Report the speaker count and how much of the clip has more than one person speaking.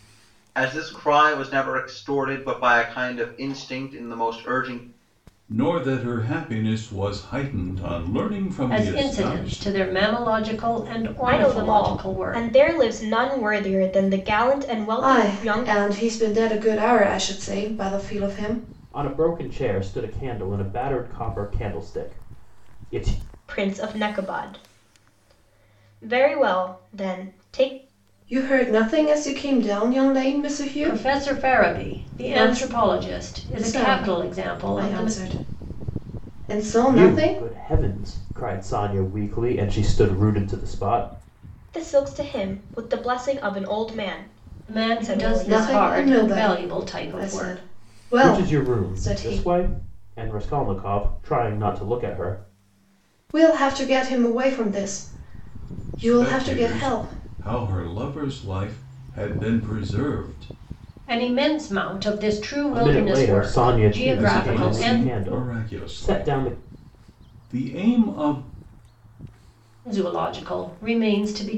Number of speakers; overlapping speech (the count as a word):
six, about 24%